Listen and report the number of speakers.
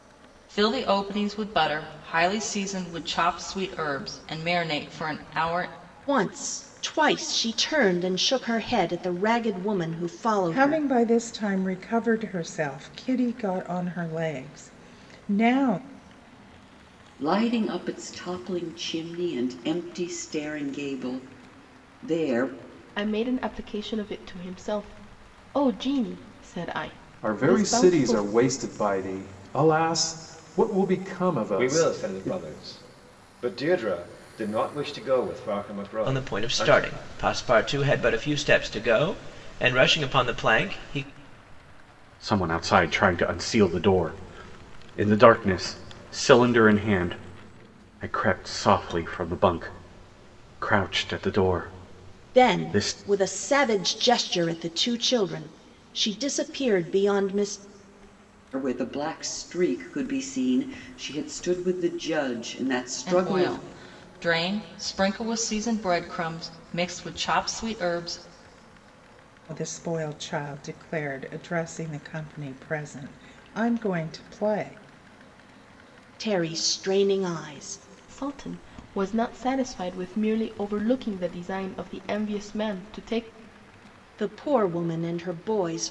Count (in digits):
9